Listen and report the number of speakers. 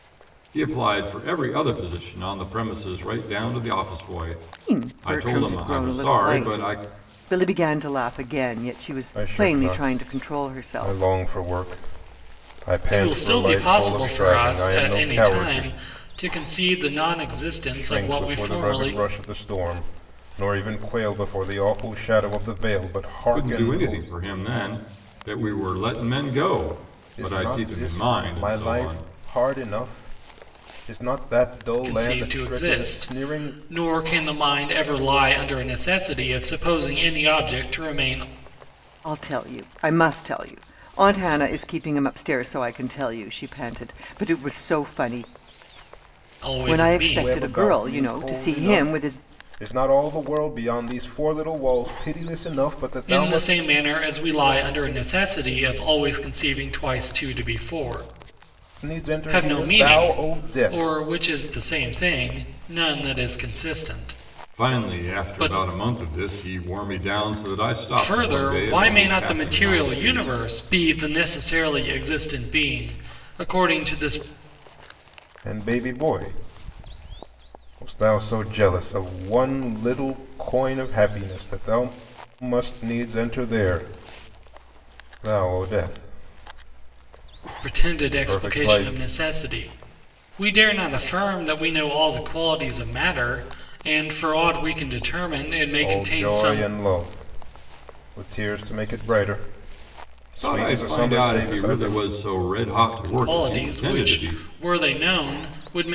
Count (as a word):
four